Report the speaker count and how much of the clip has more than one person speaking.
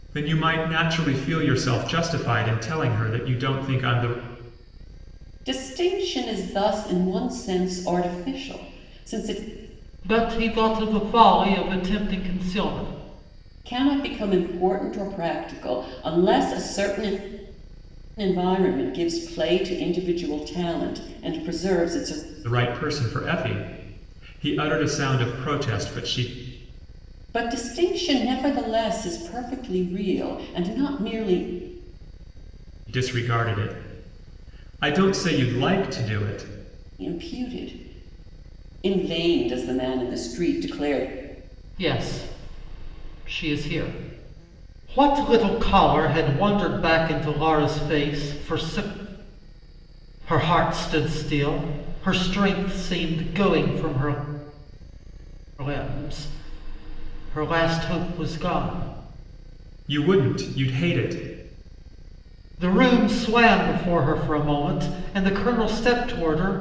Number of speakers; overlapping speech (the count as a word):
three, no overlap